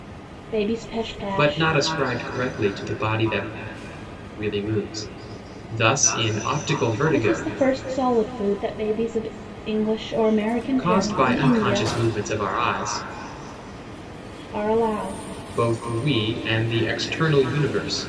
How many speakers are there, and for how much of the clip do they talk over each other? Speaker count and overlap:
2, about 11%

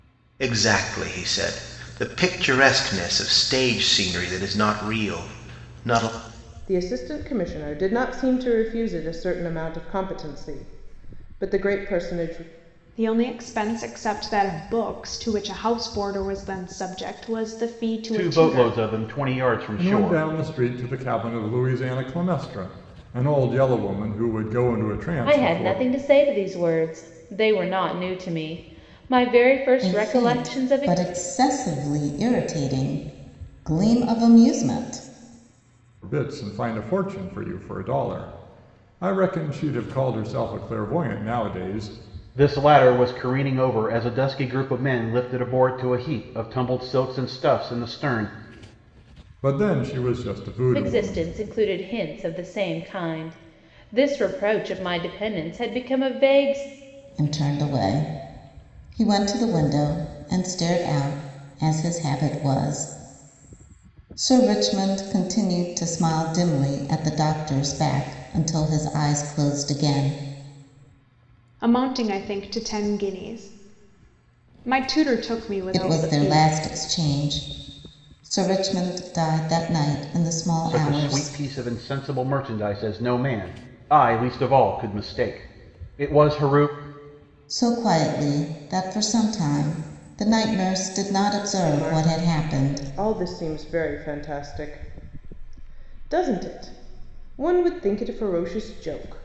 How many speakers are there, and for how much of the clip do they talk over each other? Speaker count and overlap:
7, about 6%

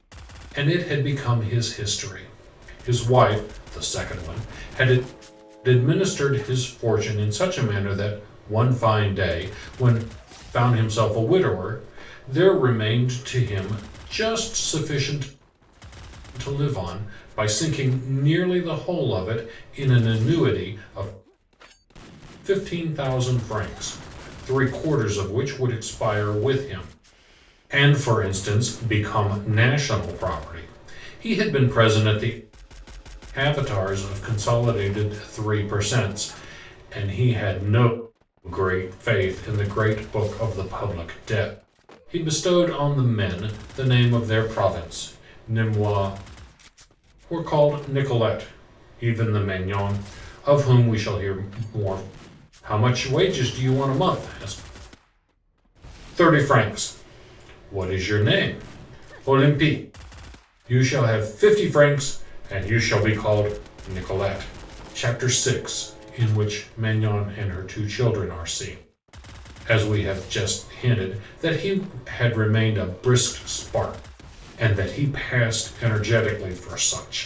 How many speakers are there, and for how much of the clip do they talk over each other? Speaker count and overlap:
1, no overlap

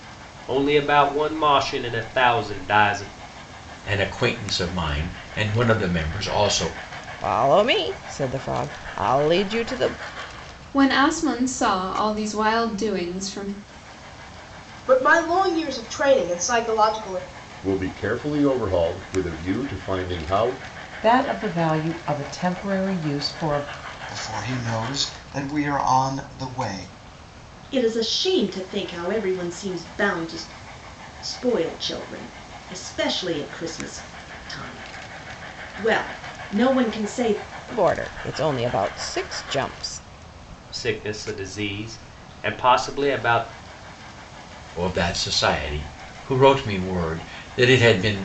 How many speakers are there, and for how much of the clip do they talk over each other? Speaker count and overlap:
9, no overlap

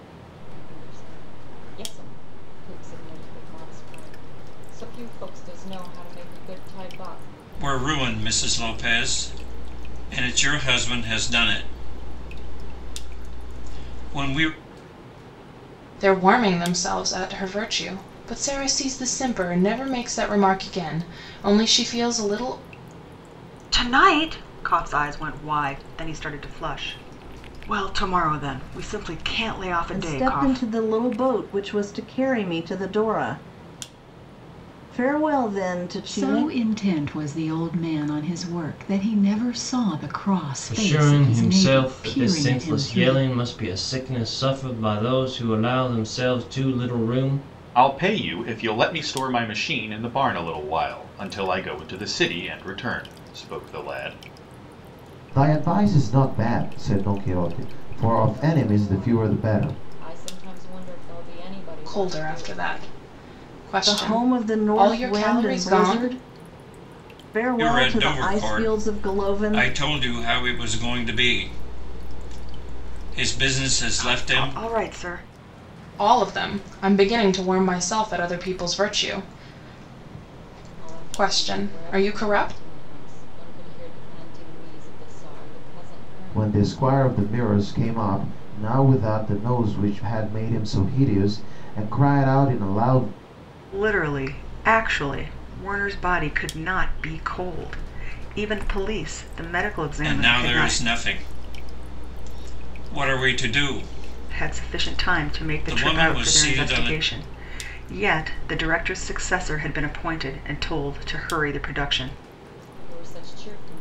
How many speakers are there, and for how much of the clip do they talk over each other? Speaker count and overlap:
9, about 16%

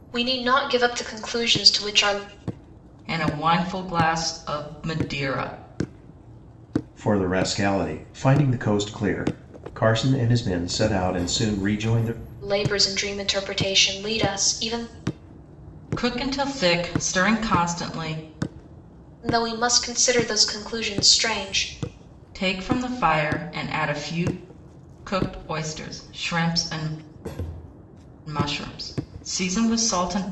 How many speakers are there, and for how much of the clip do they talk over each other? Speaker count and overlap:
3, no overlap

